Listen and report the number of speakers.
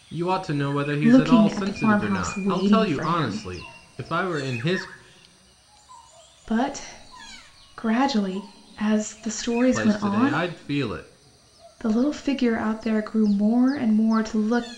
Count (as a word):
two